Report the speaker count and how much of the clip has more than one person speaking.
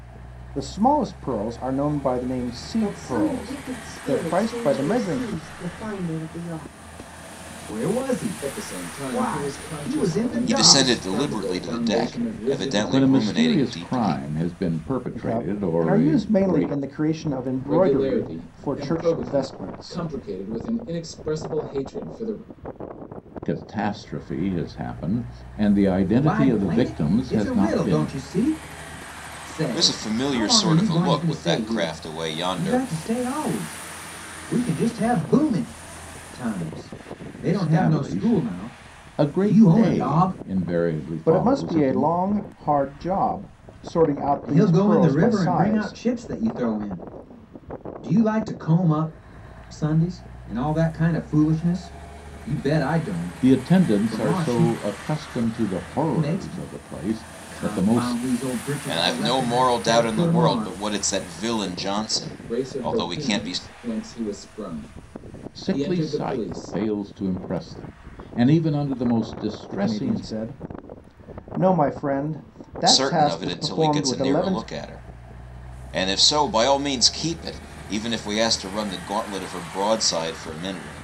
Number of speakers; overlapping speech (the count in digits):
6, about 41%